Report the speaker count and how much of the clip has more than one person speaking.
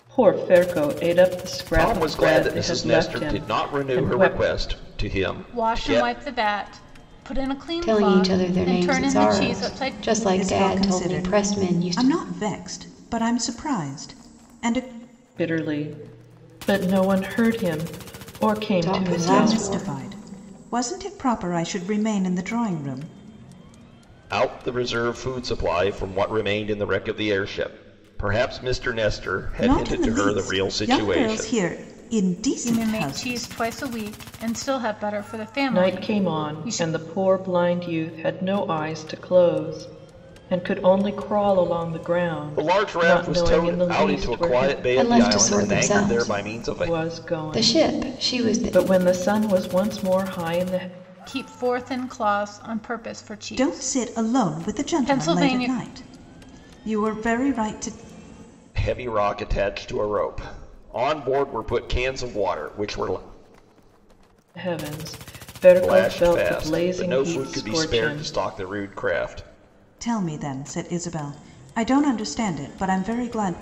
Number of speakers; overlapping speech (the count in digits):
5, about 33%